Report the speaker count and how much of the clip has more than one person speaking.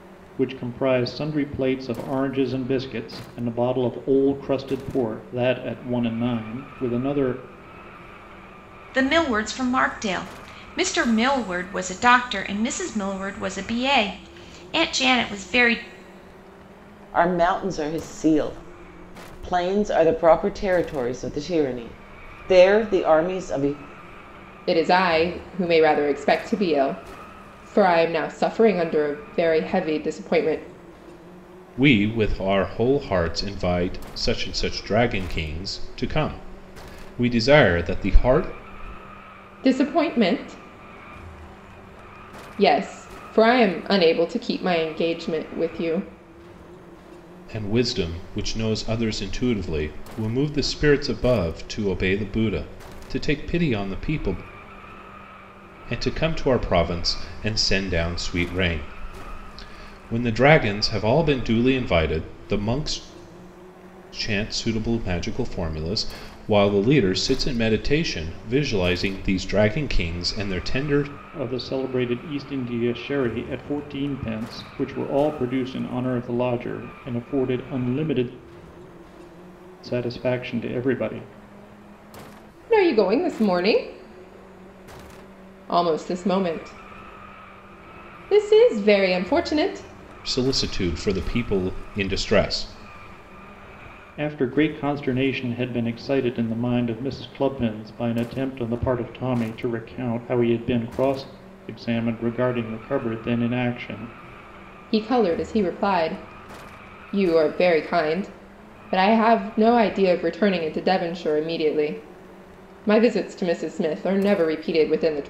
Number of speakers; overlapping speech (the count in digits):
5, no overlap